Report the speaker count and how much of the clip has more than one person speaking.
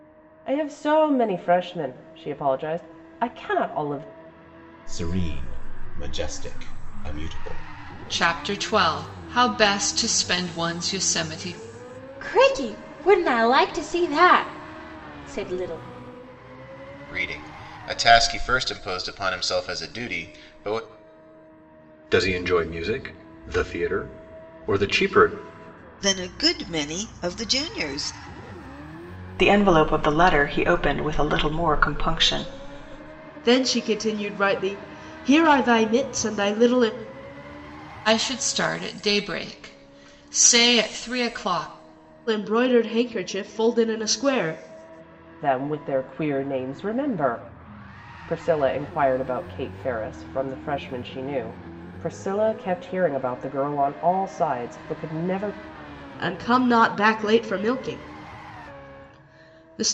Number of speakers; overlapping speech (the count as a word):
nine, no overlap